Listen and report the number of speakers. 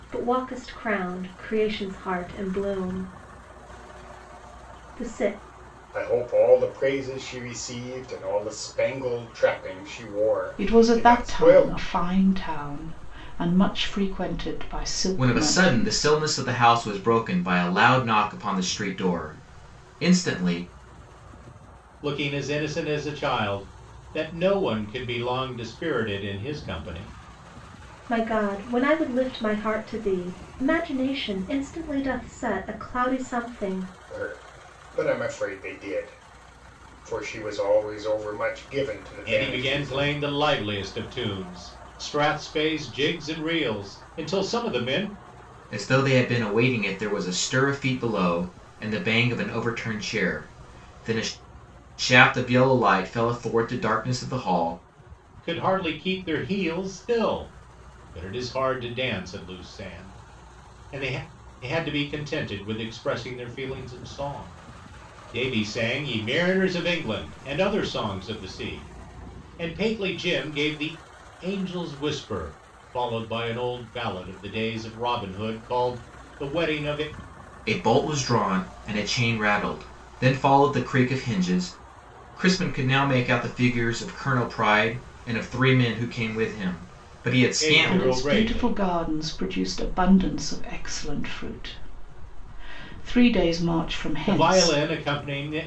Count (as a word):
five